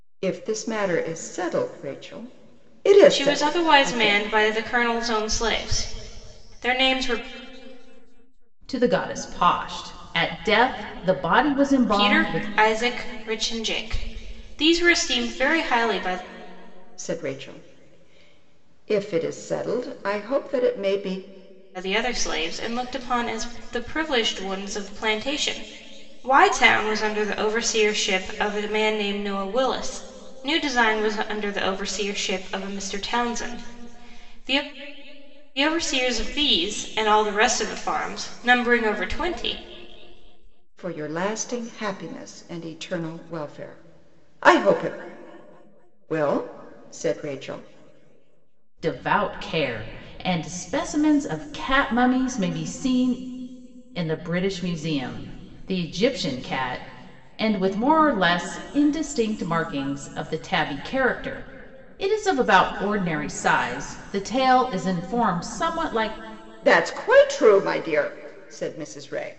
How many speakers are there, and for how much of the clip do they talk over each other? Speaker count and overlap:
3, about 3%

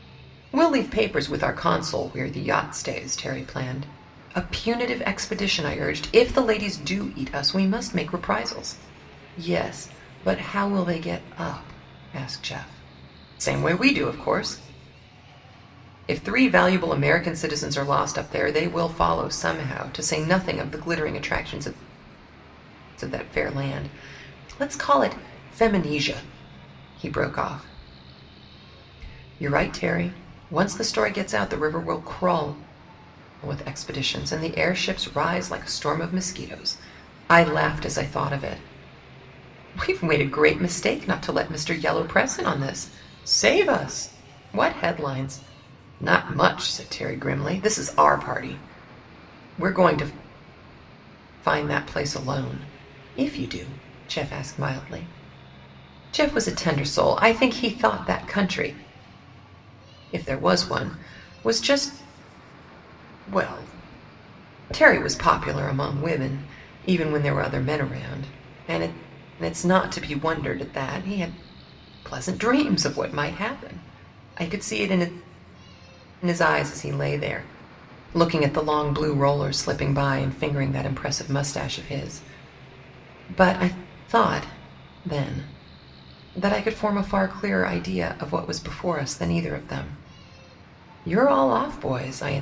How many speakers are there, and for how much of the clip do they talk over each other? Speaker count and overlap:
1, no overlap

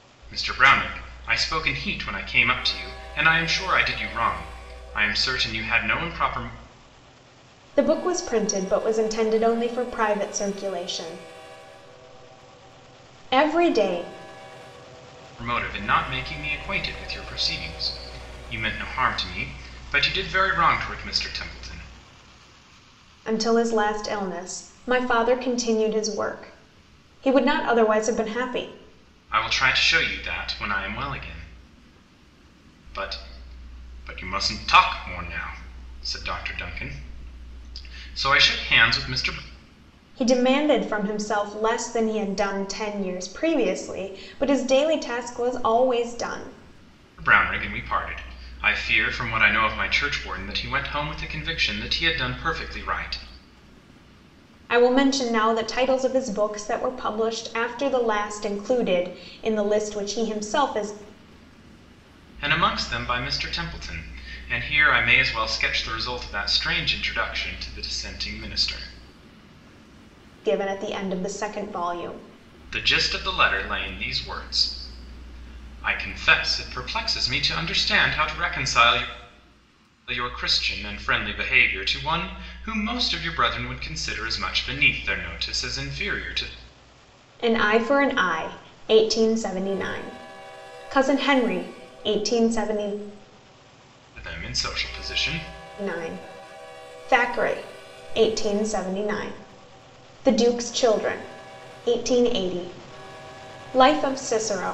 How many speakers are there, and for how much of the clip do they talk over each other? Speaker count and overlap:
2, no overlap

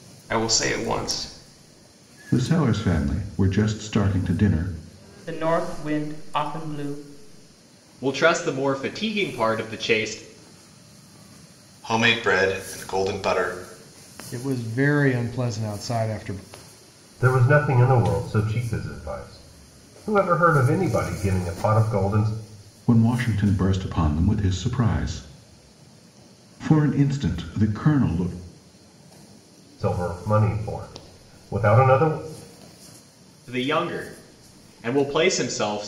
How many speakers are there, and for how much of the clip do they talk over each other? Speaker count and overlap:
7, no overlap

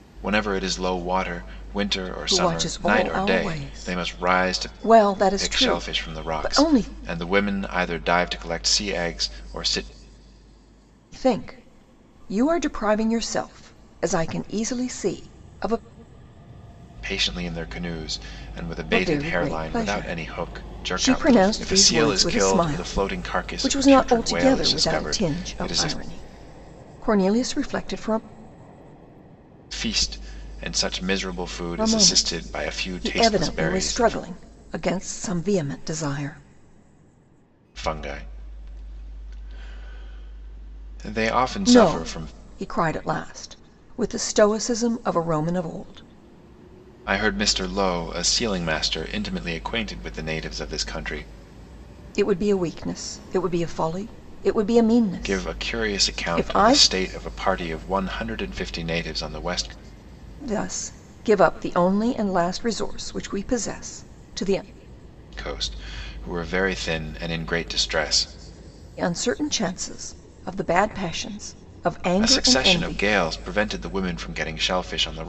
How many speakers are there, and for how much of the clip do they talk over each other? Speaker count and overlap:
2, about 22%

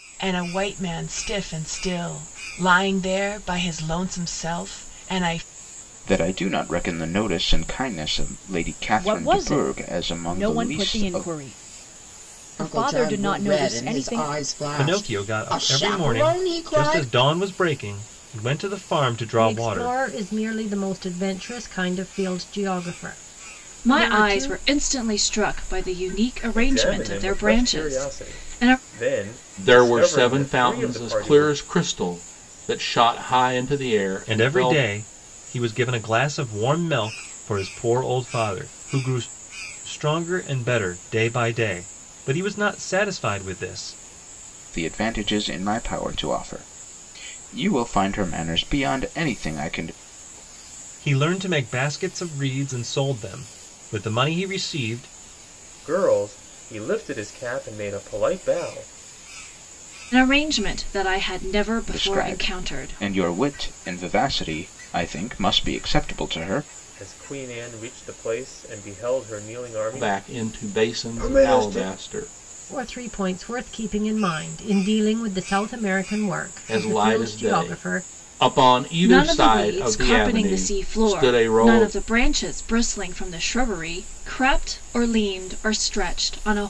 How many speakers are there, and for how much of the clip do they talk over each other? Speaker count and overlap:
9, about 23%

